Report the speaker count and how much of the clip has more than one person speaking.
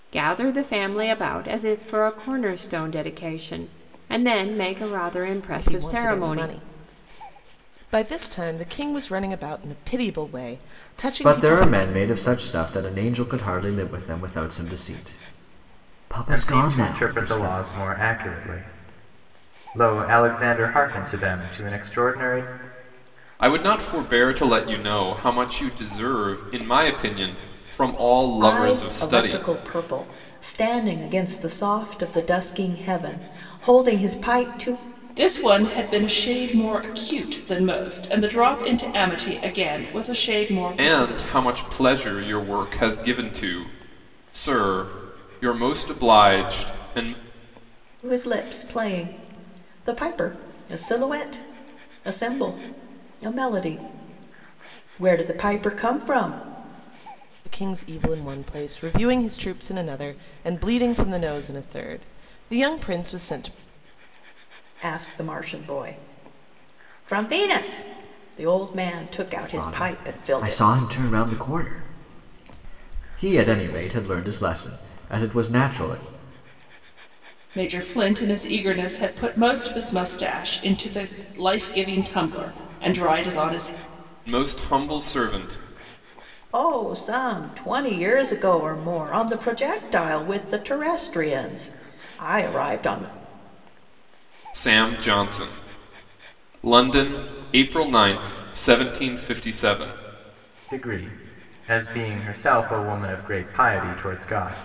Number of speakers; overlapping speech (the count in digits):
7, about 6%